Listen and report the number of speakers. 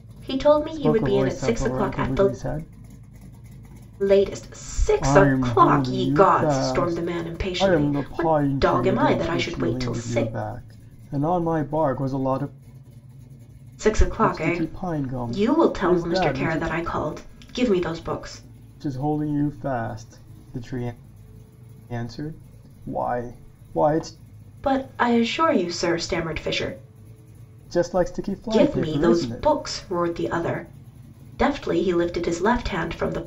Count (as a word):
two